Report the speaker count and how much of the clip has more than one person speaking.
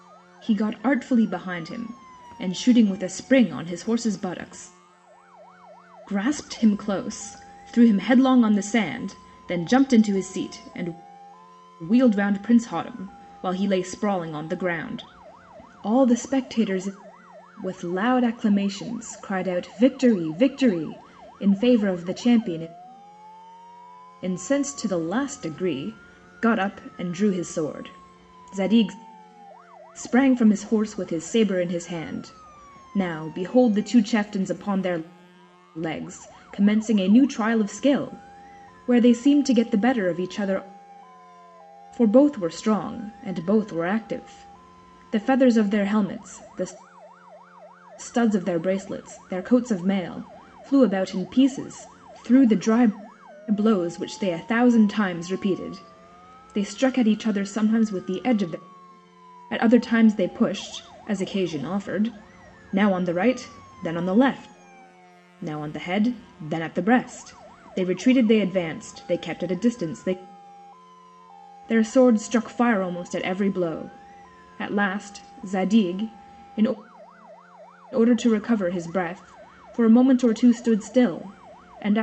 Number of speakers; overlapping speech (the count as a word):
one, no overlap